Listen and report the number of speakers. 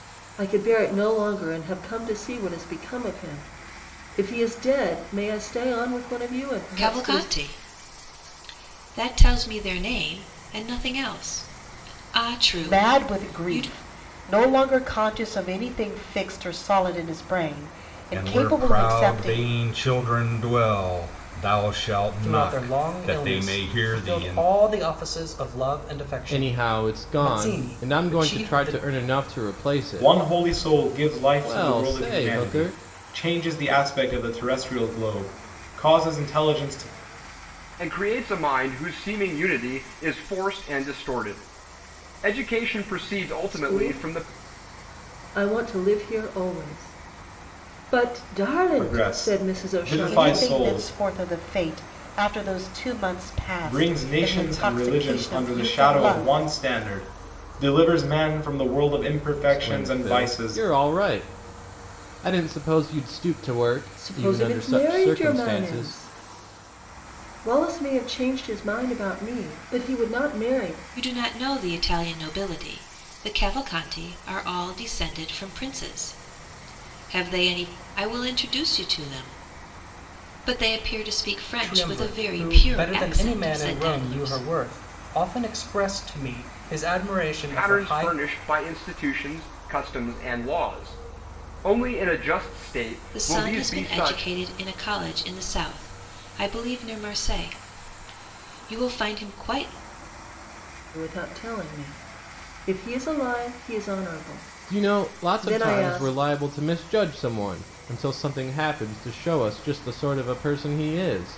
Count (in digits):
8